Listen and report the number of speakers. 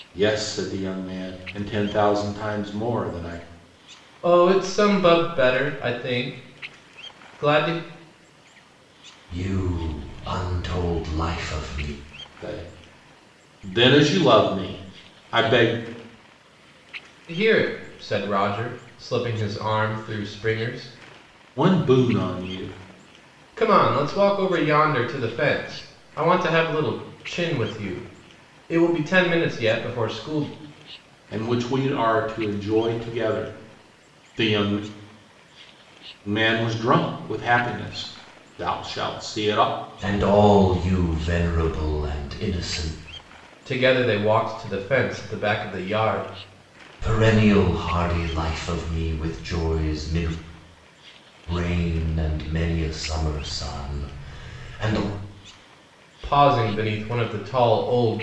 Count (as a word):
three